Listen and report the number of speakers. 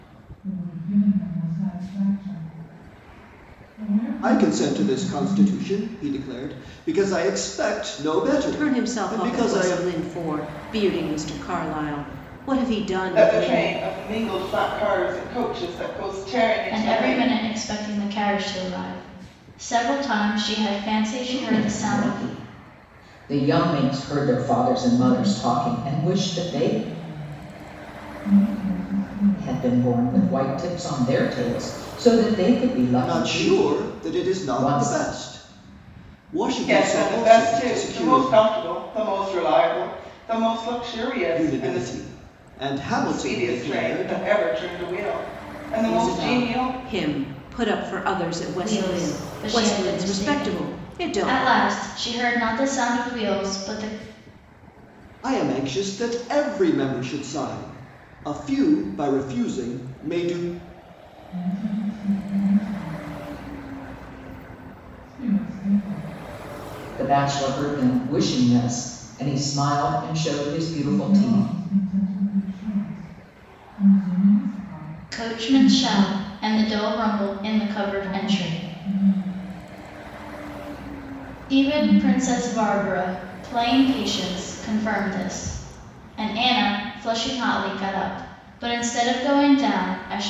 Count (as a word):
six